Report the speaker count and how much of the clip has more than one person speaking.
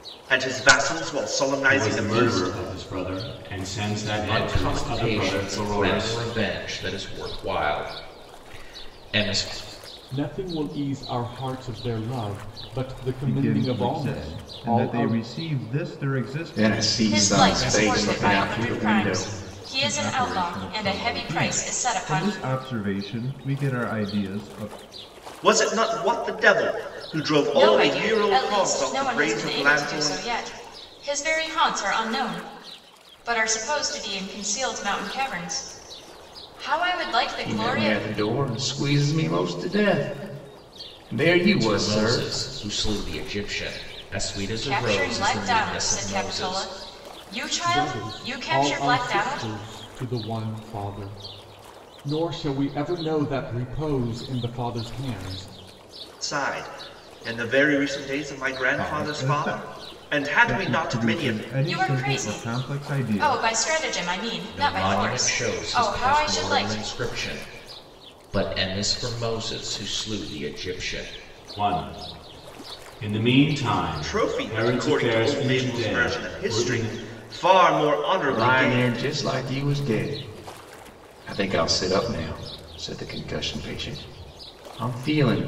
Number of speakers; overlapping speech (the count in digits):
7, about 34%